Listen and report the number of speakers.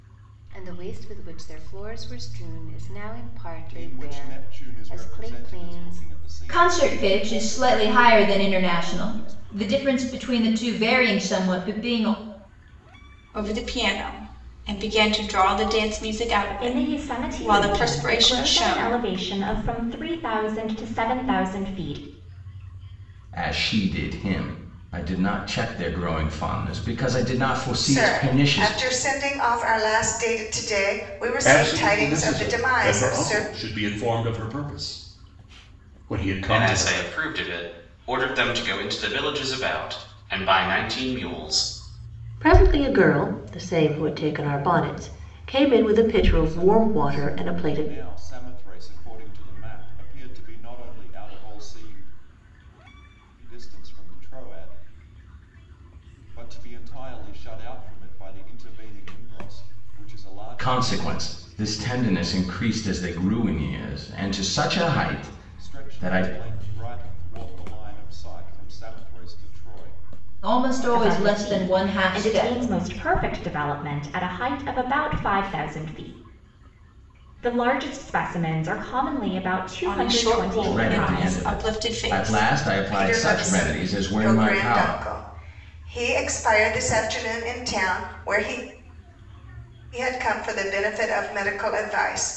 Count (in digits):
10